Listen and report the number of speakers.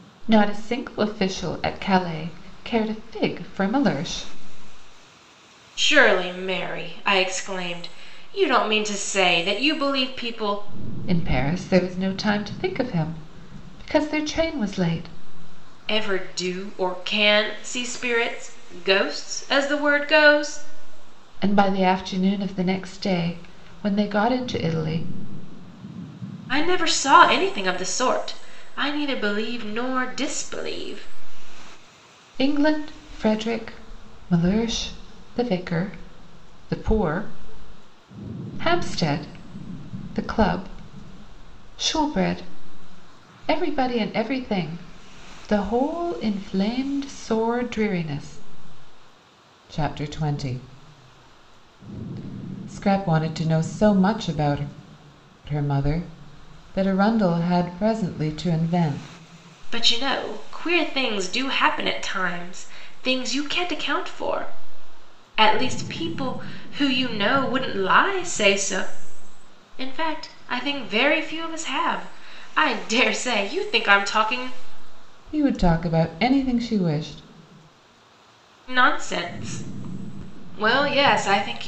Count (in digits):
2